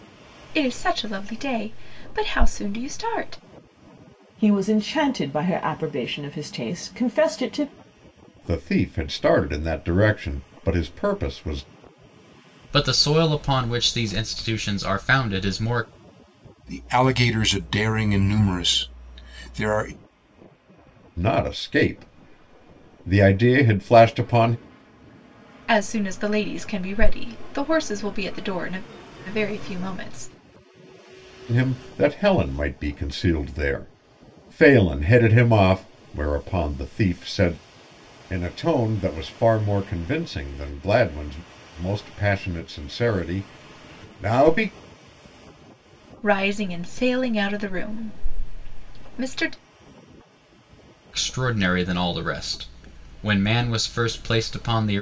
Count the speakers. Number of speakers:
5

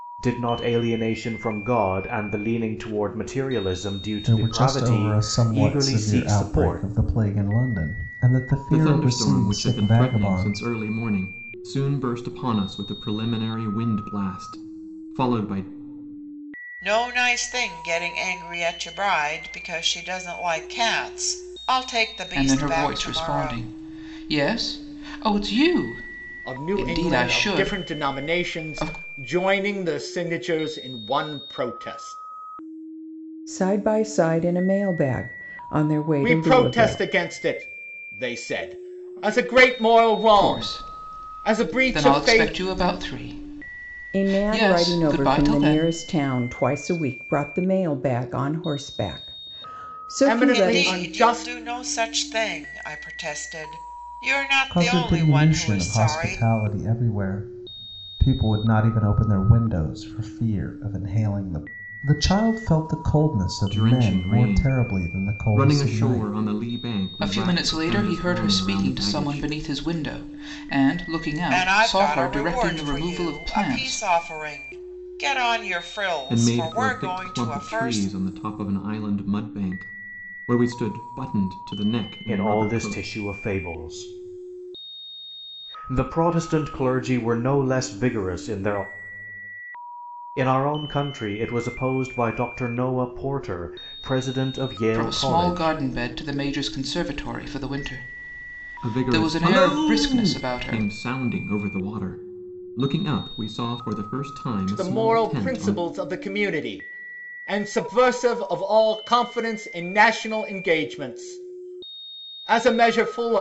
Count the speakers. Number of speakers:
7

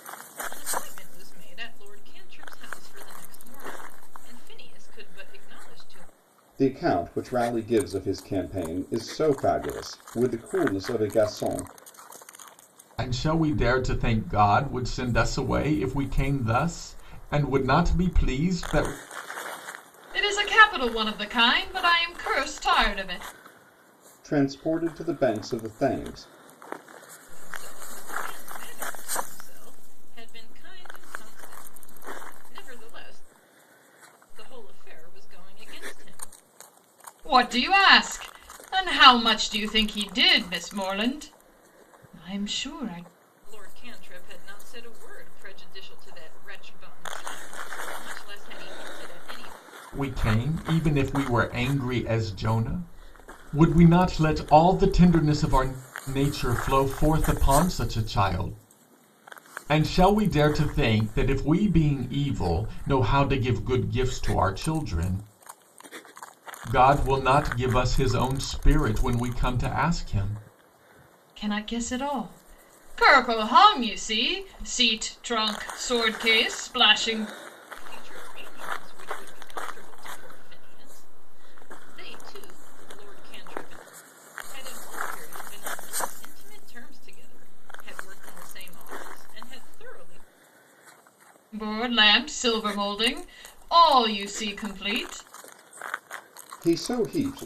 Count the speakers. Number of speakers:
4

